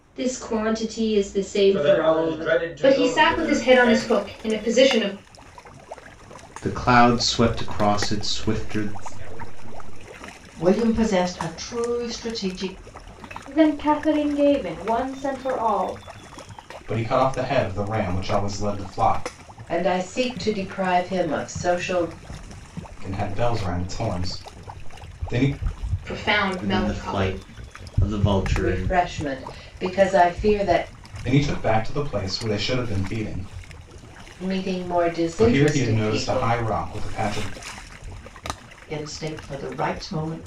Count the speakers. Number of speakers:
9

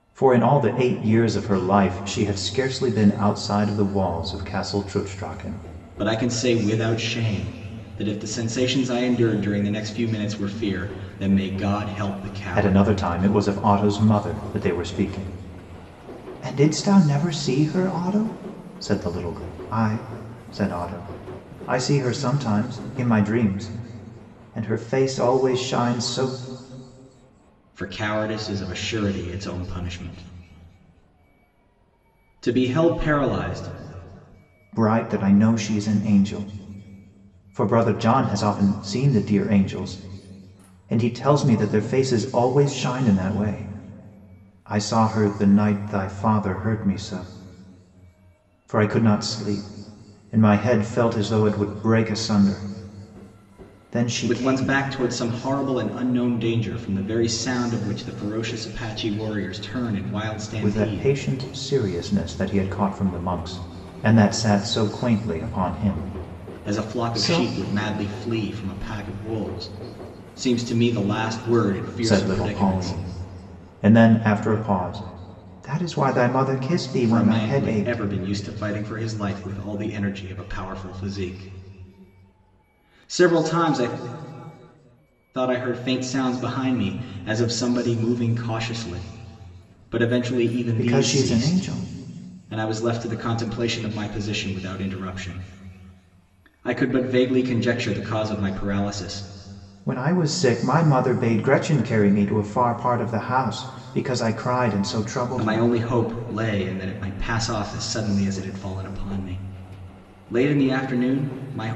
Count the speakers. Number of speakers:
2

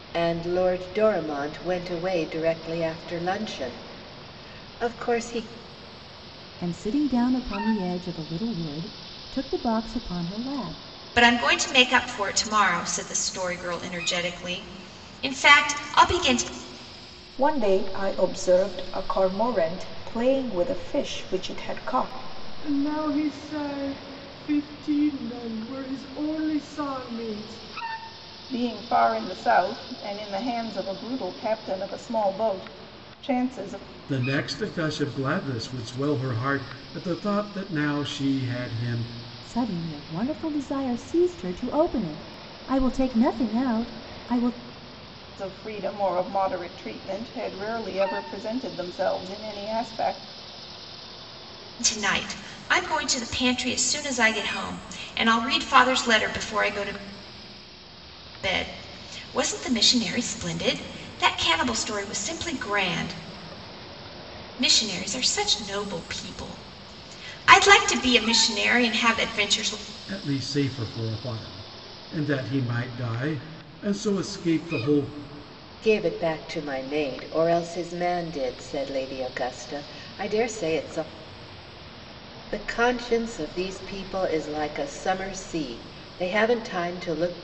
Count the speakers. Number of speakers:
7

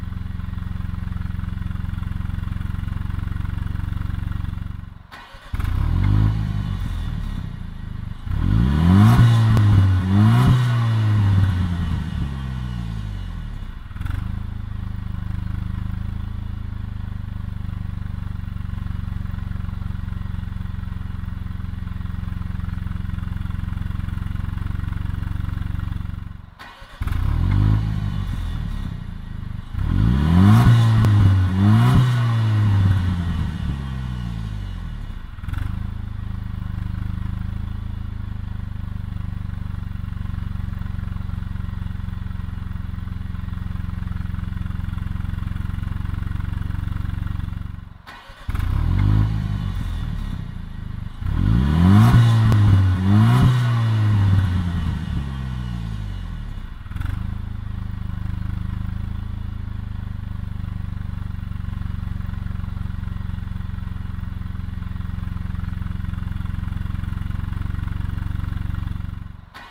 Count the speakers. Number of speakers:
0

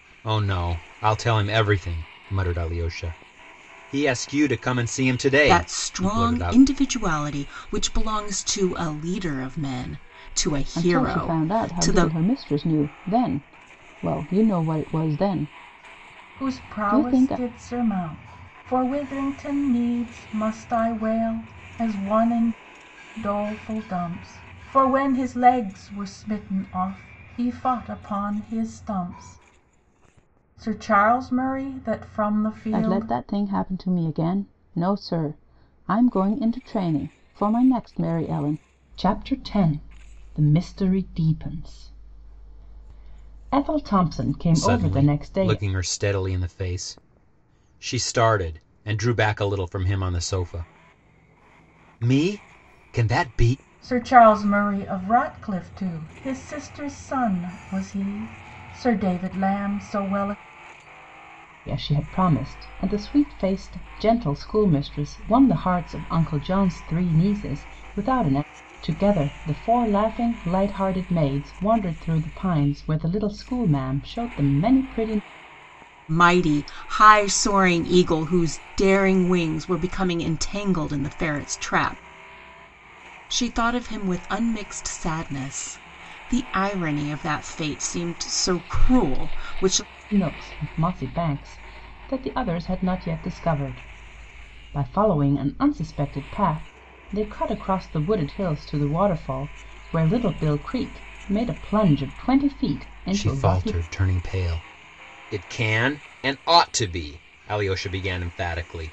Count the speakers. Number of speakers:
4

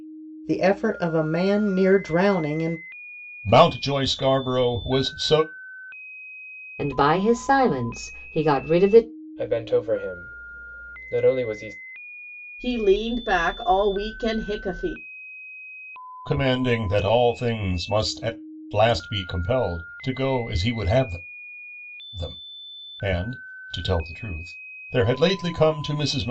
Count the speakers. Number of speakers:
5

